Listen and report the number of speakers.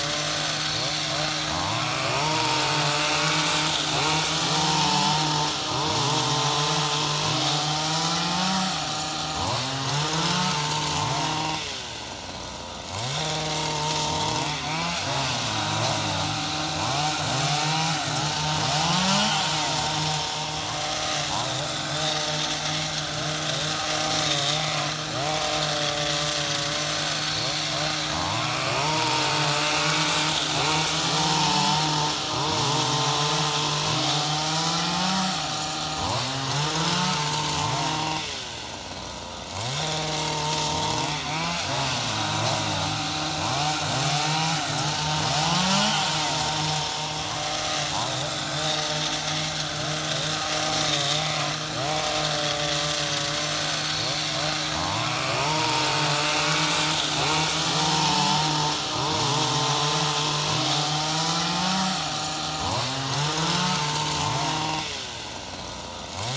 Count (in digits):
0